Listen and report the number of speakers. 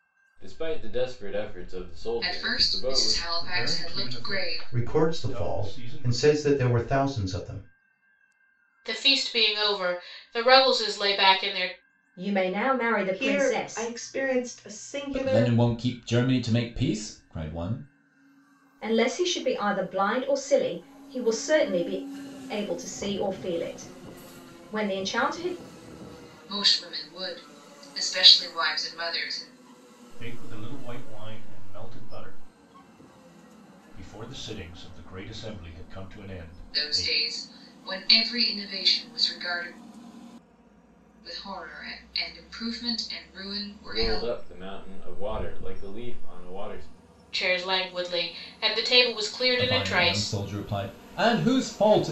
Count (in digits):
8